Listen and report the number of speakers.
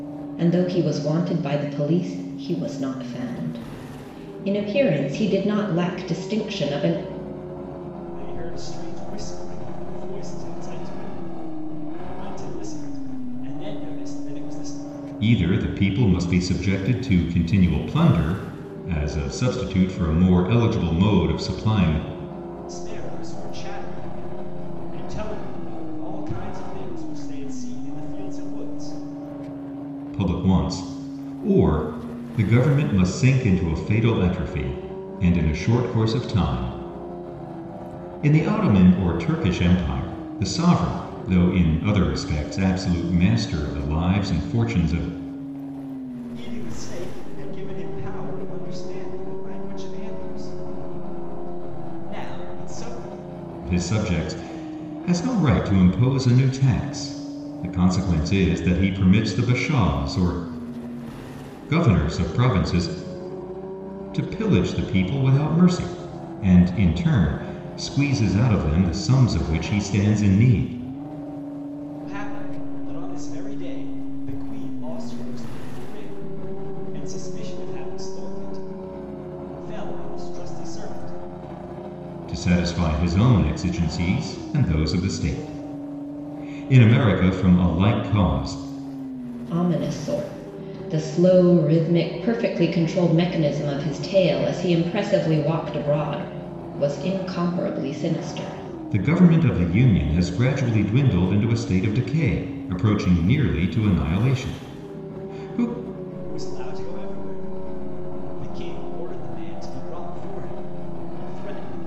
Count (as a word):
three